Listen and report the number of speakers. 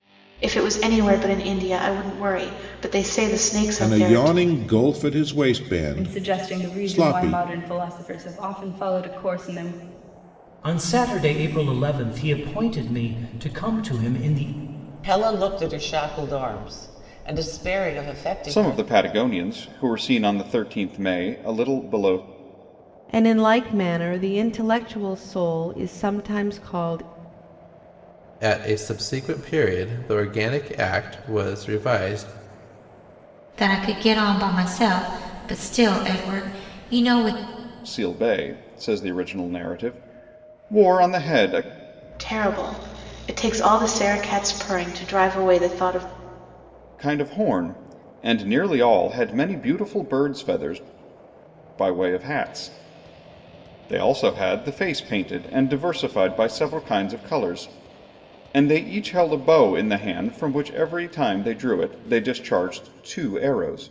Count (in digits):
9